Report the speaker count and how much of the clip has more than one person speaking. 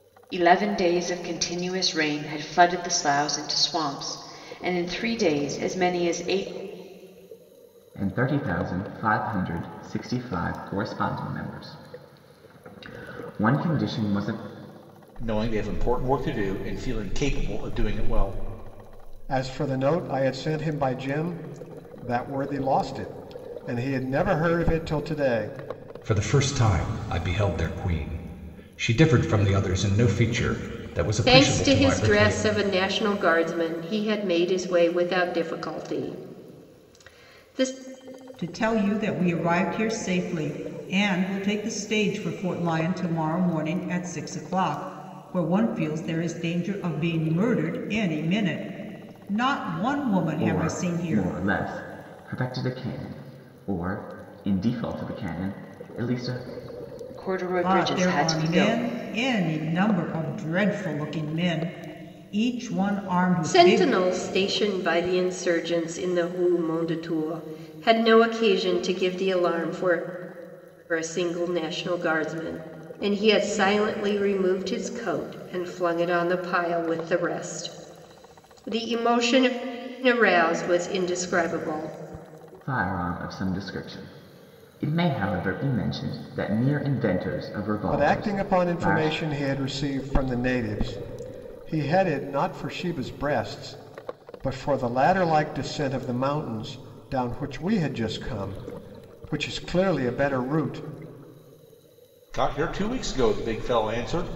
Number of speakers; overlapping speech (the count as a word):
seven, about 5%